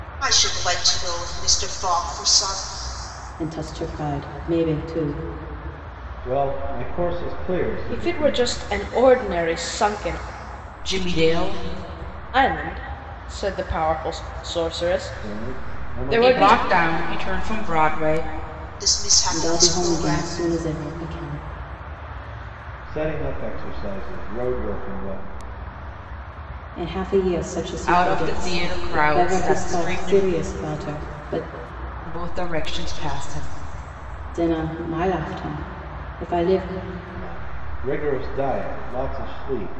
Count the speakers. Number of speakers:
5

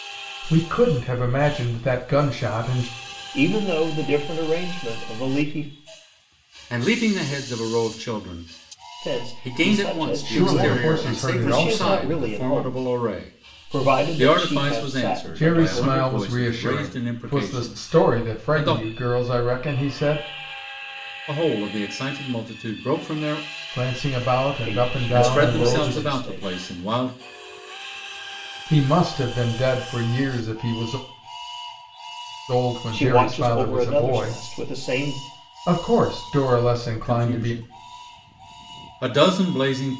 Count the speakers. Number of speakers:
3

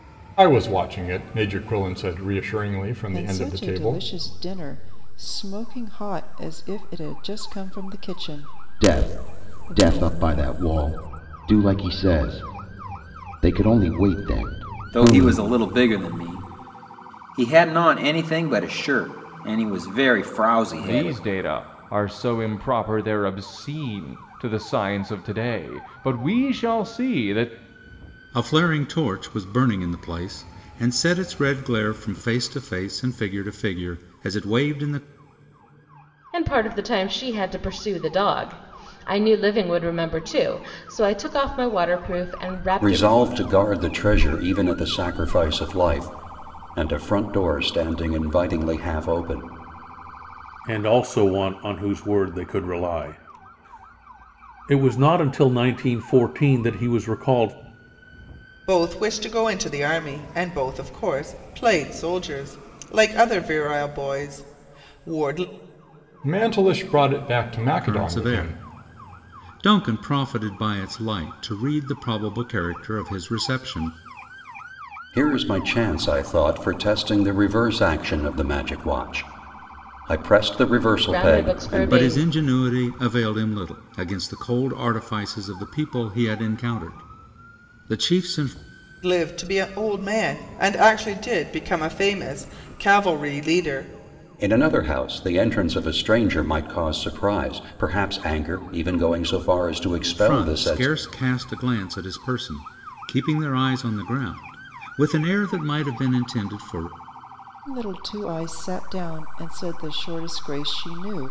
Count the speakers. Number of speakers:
10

